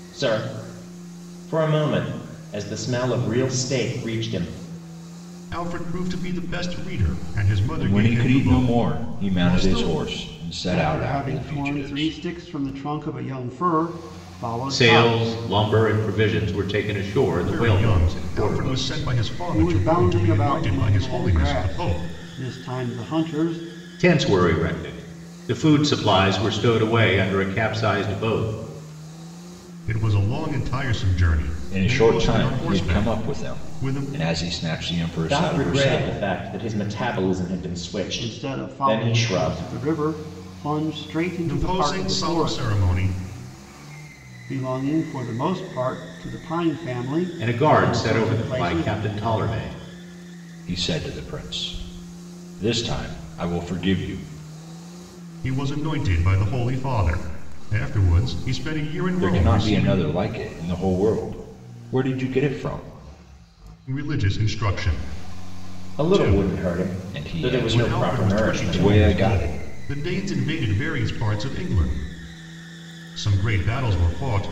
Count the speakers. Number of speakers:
5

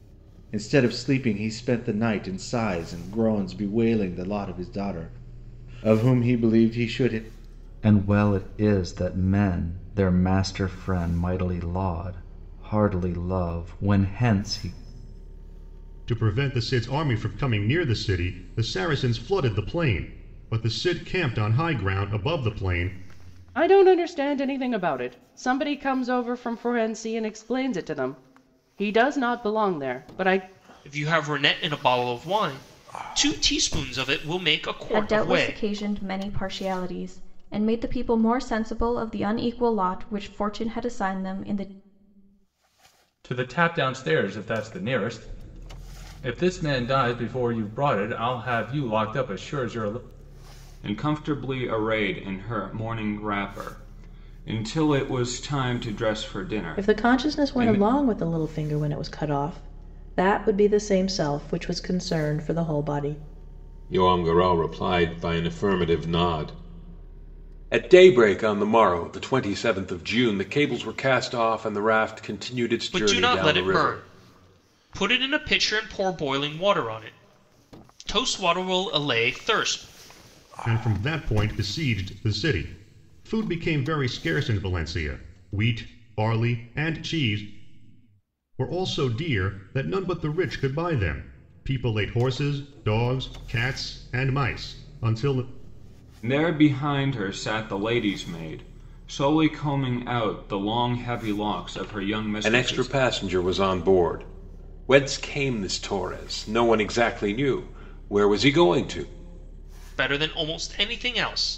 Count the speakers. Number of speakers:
10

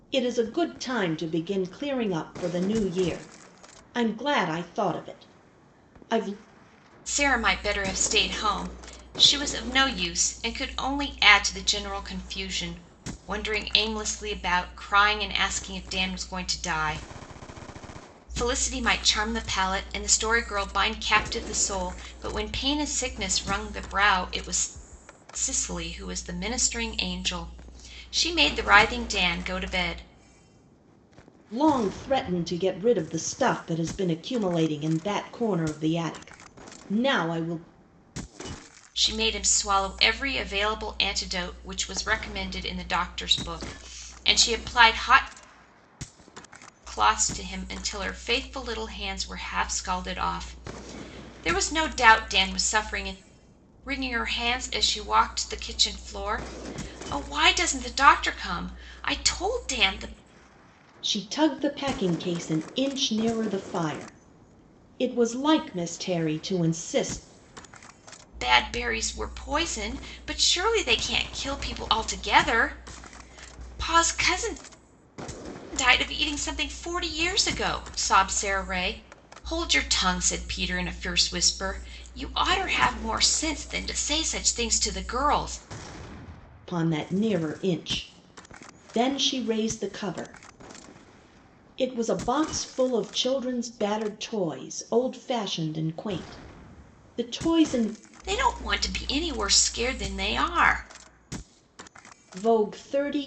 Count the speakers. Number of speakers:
2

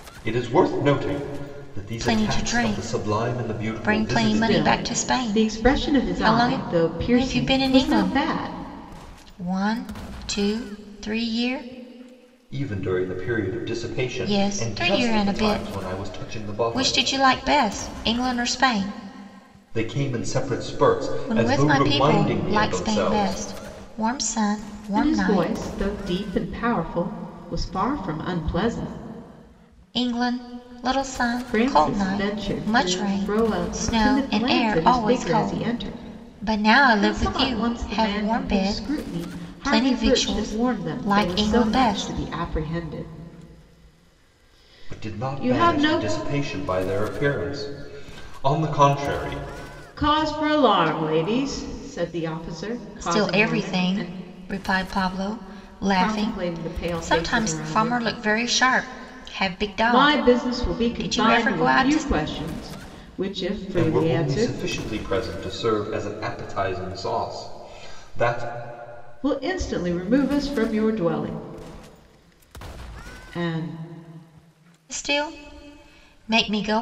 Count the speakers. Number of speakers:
3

